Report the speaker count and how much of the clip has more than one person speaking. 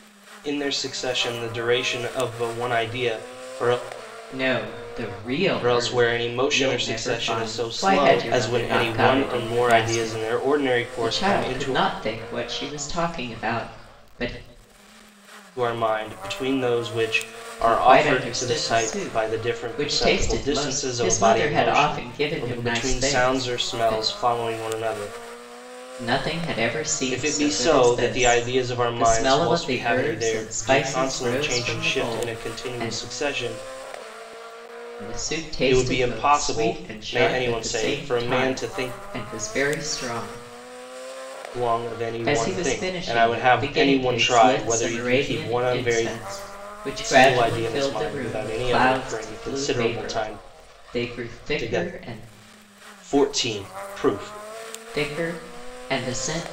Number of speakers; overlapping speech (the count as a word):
two, about 52%